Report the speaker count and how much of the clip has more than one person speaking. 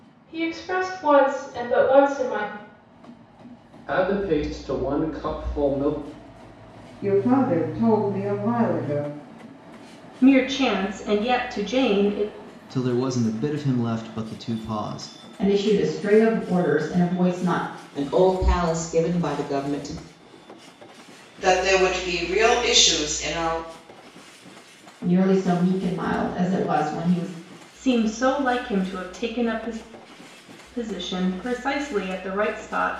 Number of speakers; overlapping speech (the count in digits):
8, no overlap